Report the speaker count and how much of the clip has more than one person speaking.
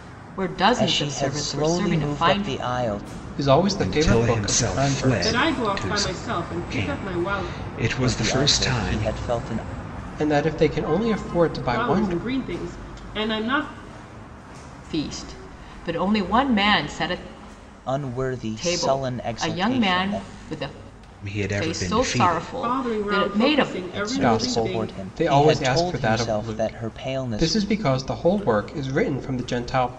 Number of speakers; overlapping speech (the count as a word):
five, about 49%